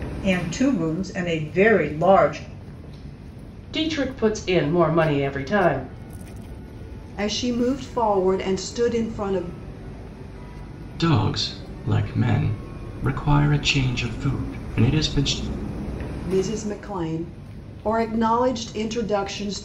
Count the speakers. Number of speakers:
4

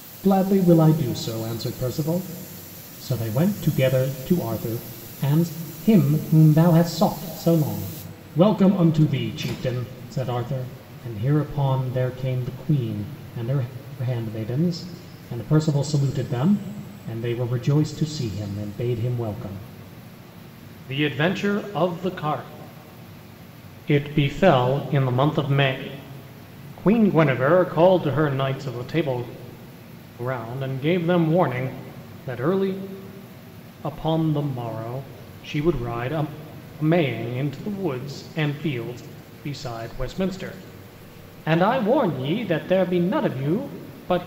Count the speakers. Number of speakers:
1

